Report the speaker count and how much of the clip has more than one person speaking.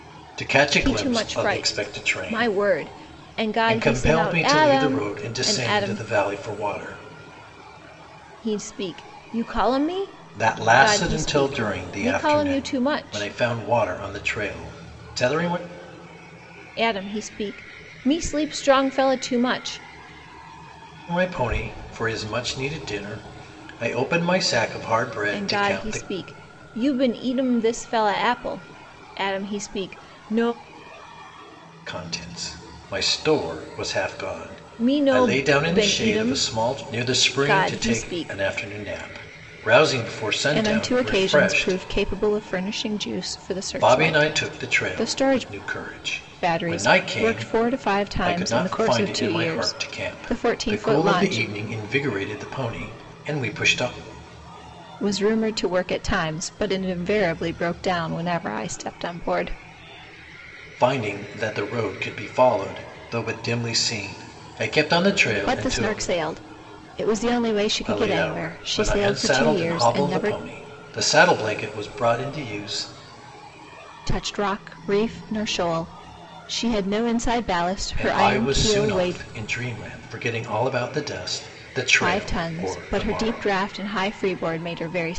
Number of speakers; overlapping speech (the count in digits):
2, about 31%